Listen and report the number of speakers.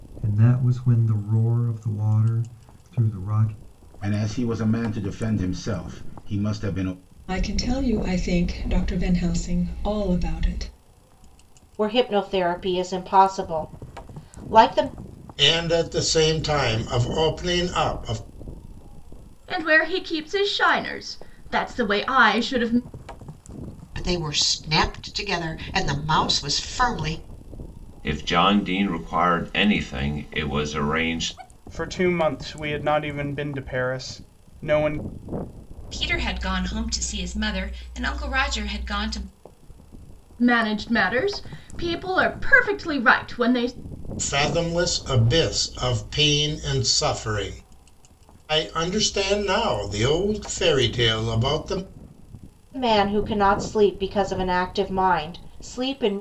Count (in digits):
10